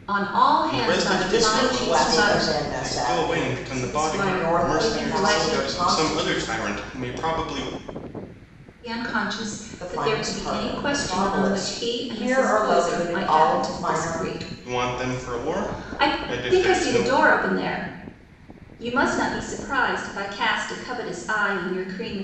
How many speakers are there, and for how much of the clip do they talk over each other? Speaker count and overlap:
3, about 54%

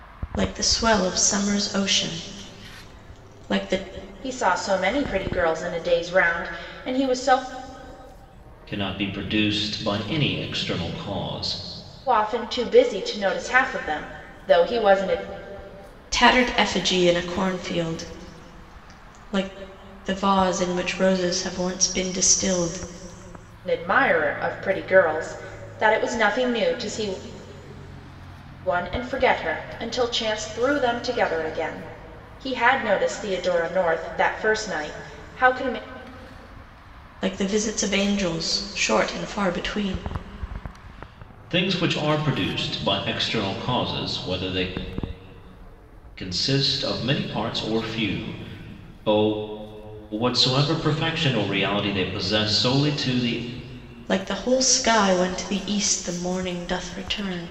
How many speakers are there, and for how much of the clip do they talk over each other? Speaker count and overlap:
3, no overlap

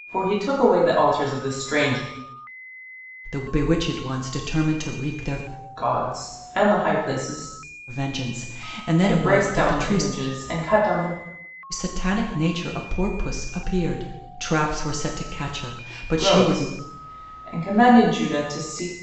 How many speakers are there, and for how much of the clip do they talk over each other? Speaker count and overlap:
2, about 9%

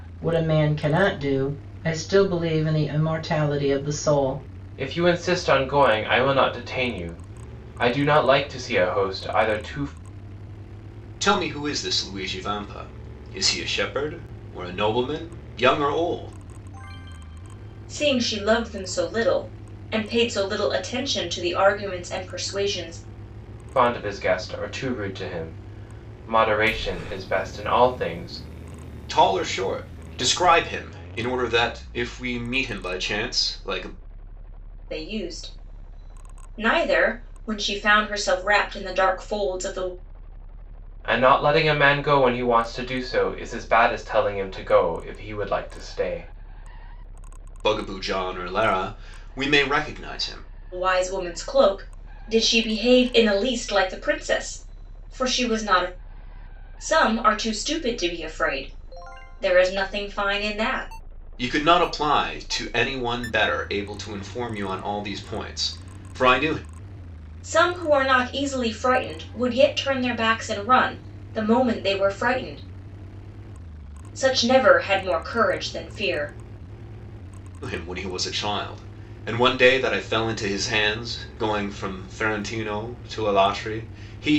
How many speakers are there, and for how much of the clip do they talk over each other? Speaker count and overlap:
4, no overlap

